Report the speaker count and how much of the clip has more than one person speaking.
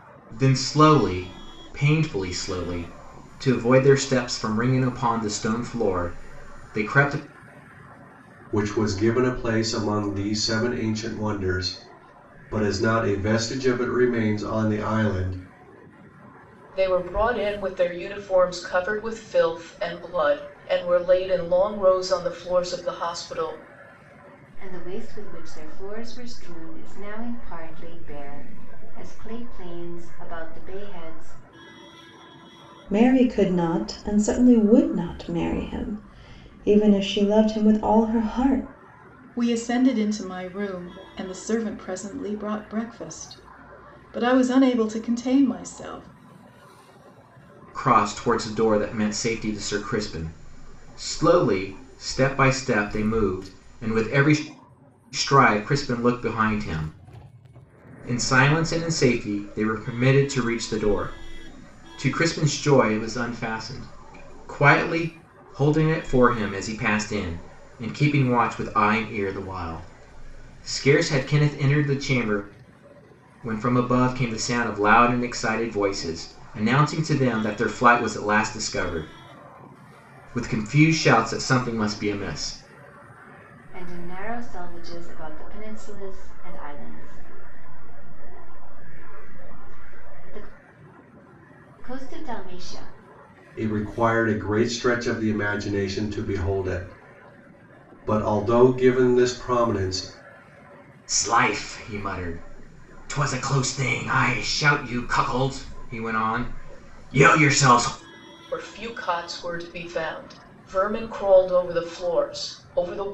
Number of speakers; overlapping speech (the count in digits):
6, no overlap